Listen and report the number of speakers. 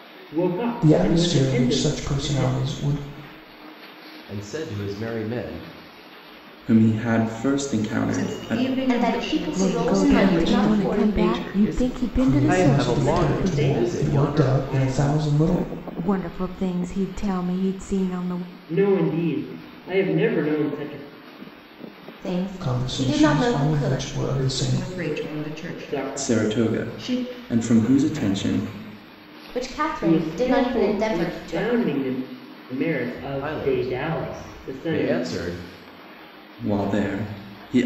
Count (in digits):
8